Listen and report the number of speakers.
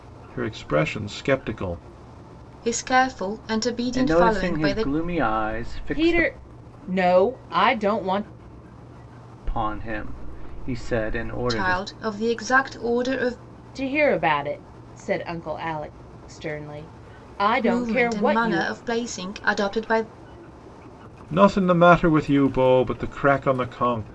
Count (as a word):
four